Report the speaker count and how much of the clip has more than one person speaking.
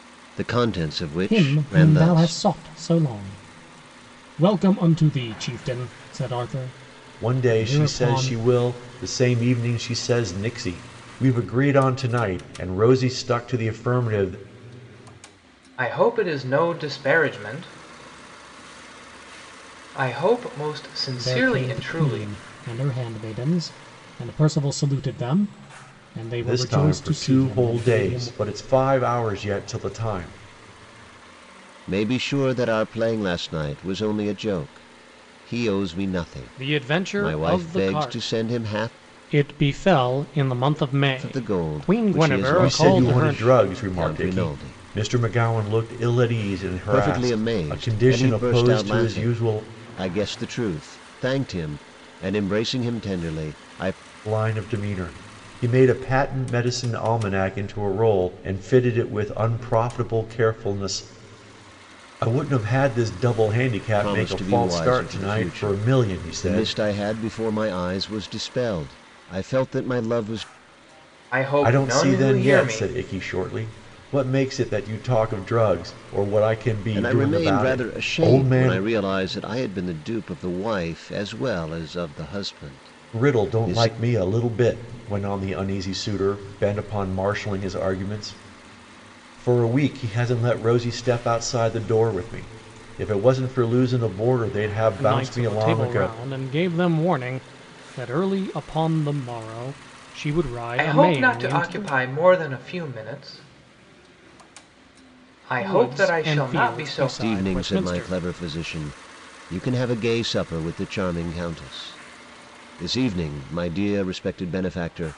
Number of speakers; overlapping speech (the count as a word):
four, about 22%